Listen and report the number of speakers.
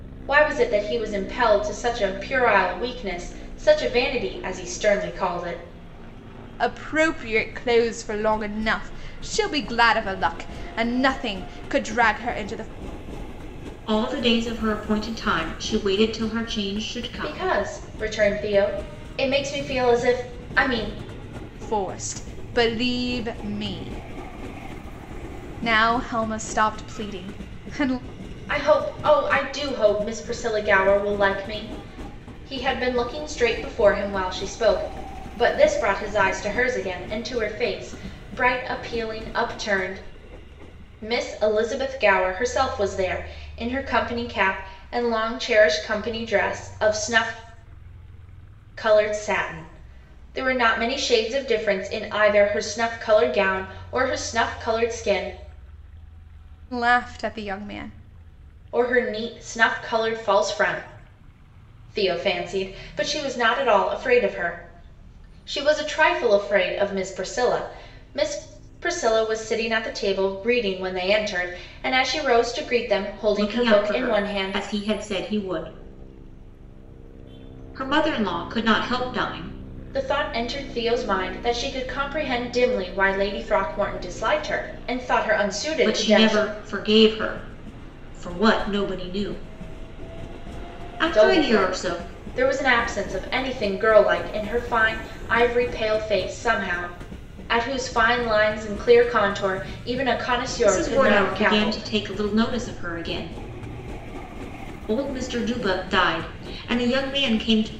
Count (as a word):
three